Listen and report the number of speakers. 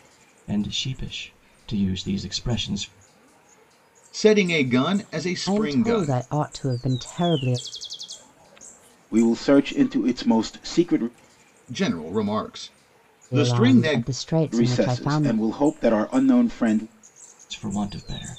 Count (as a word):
four